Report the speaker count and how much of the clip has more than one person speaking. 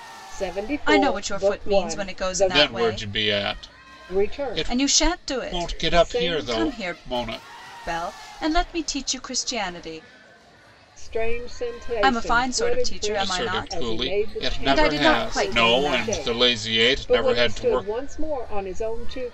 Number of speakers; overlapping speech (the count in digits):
3, about 57%